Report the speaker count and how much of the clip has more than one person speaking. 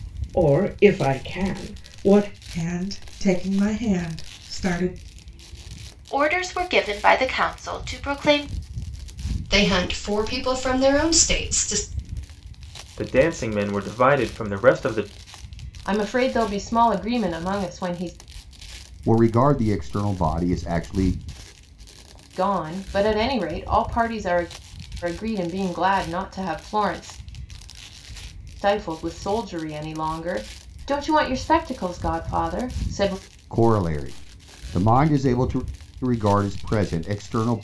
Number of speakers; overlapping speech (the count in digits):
7, no overlap